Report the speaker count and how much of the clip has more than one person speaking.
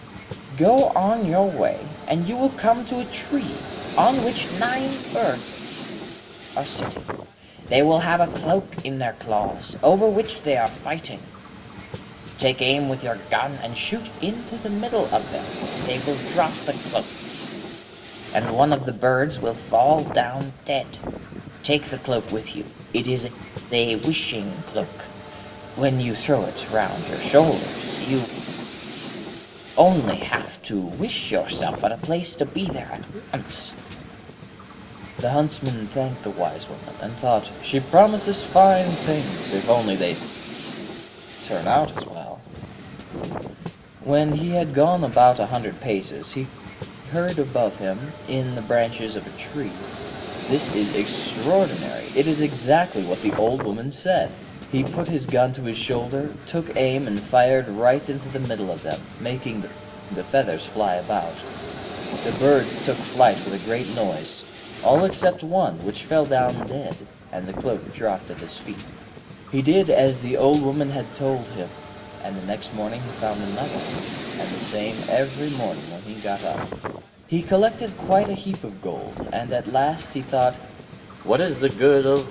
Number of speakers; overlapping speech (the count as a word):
one, no overlap